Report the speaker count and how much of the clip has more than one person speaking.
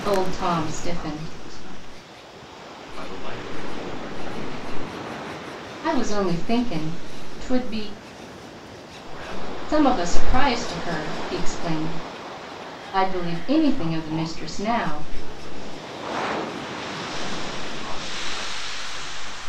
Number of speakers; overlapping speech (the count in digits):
2, about 22%